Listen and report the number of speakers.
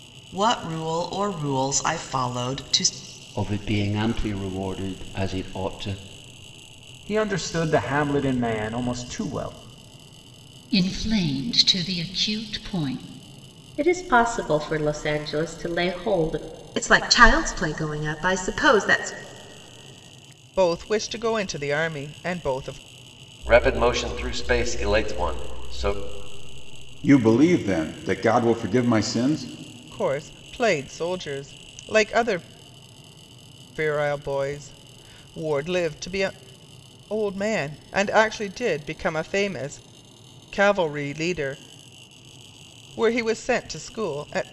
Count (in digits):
9